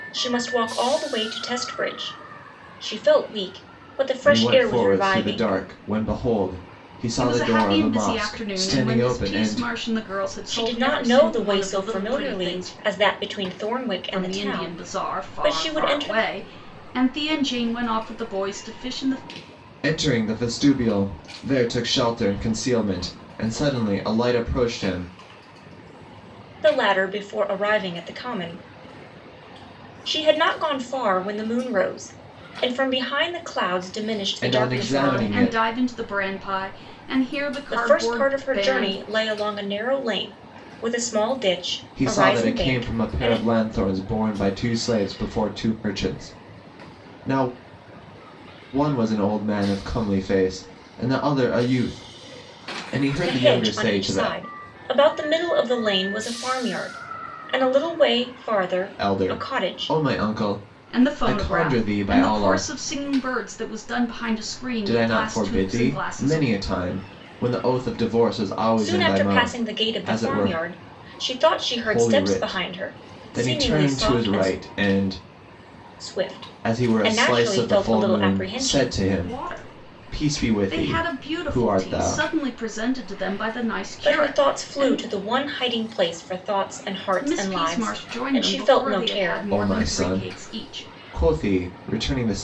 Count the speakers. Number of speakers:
3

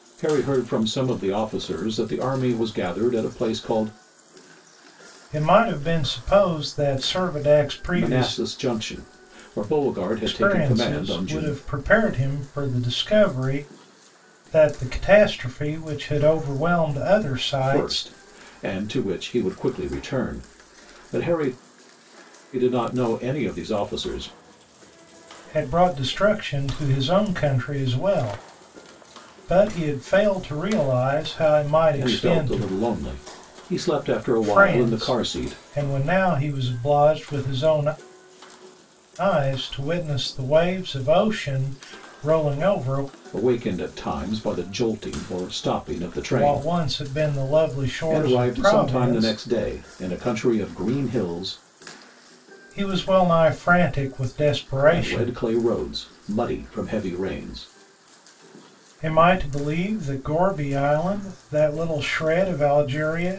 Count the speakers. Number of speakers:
2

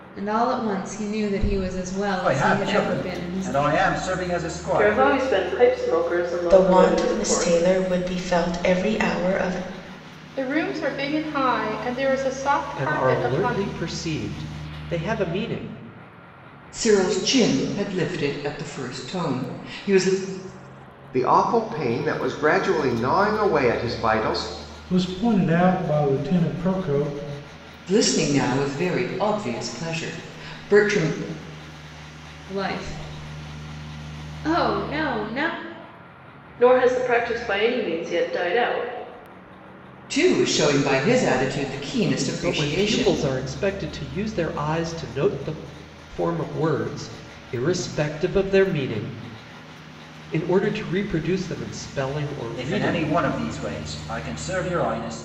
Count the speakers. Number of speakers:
9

